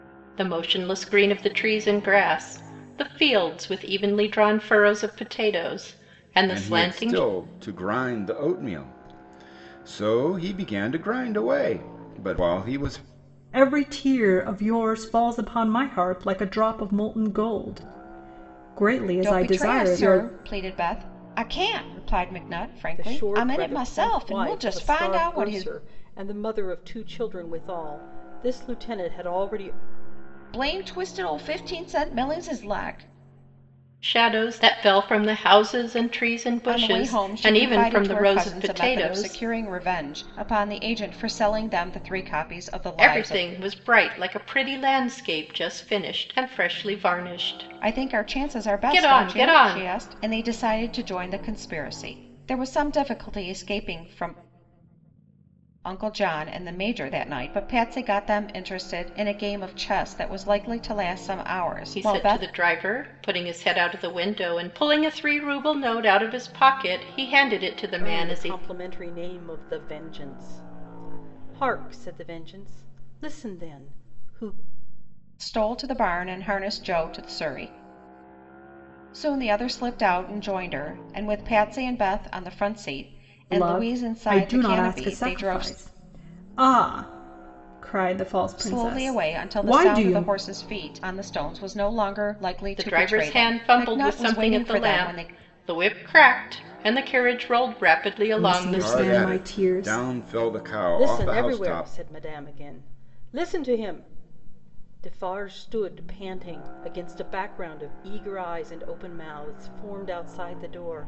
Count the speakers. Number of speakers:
5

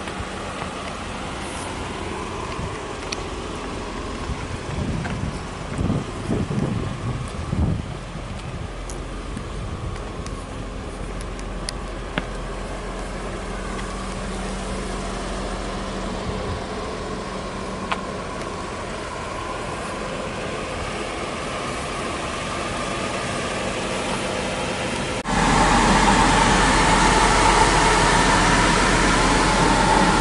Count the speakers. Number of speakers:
0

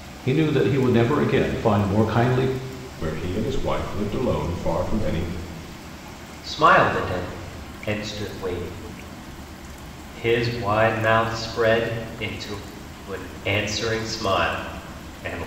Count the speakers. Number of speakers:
3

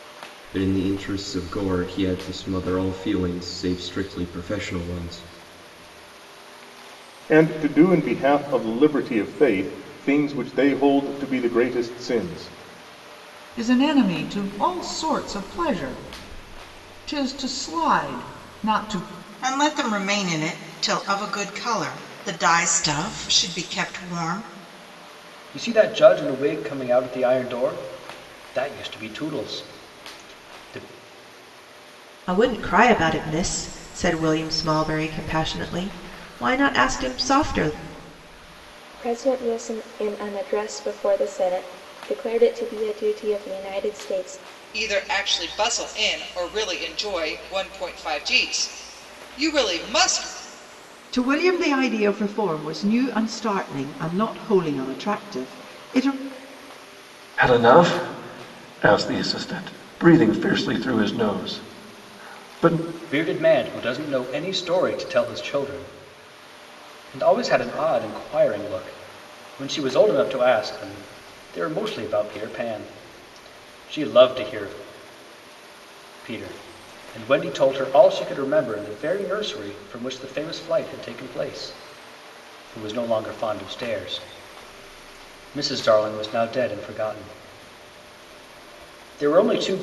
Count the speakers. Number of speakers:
10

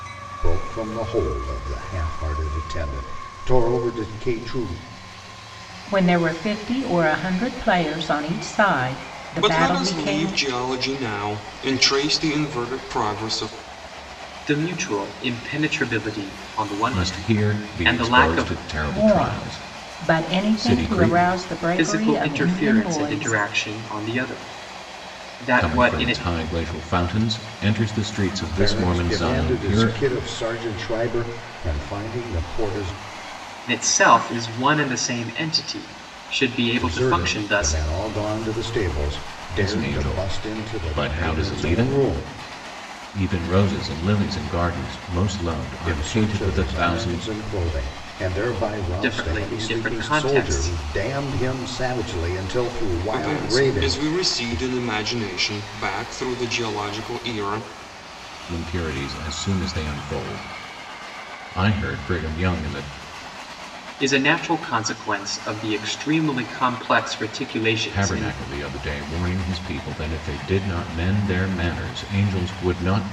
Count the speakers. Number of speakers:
5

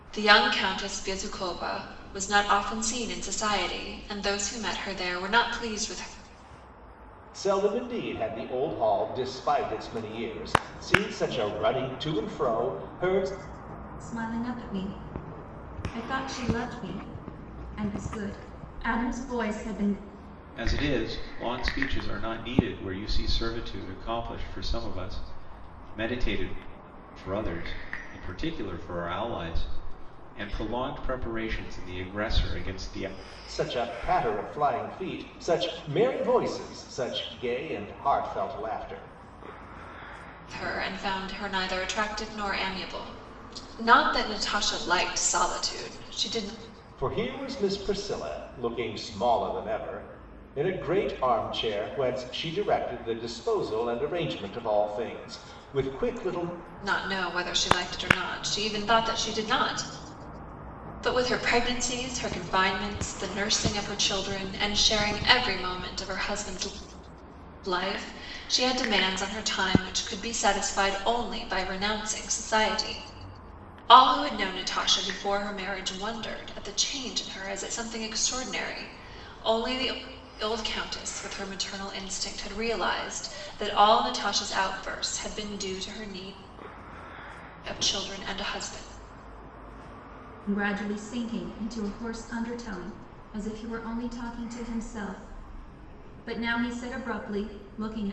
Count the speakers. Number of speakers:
4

